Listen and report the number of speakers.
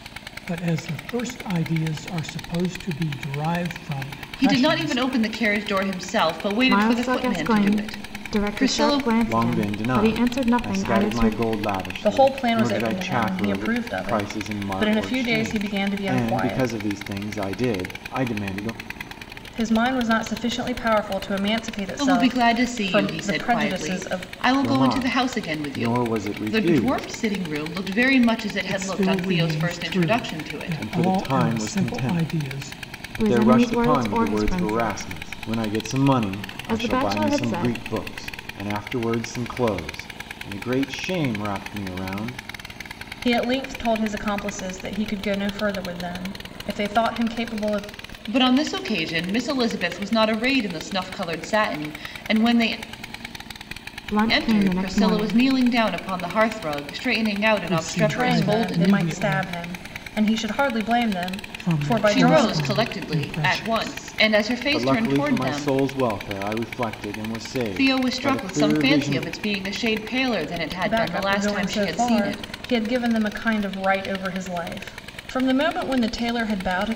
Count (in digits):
5